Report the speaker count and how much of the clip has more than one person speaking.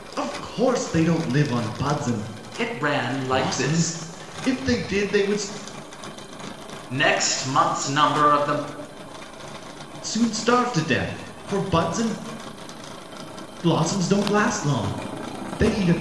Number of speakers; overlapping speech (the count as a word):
two, about 4%